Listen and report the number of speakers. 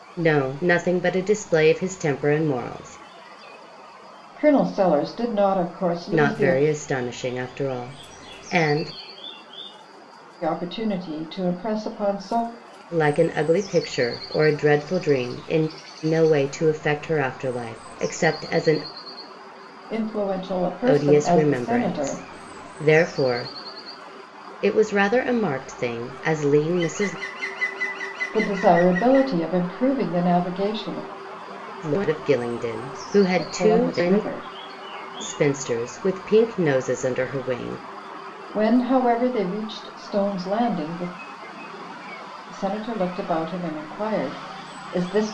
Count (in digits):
2